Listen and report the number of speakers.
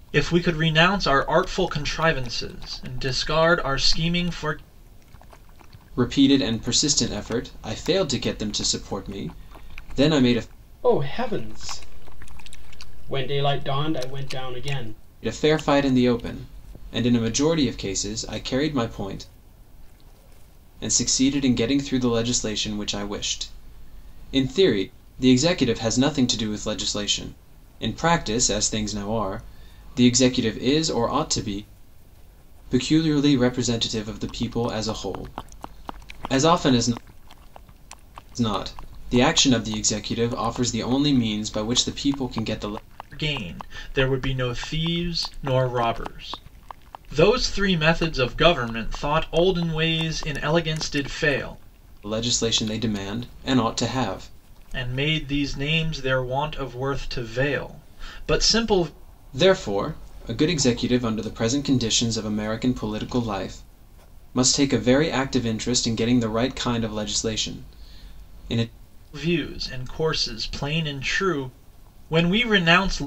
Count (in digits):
3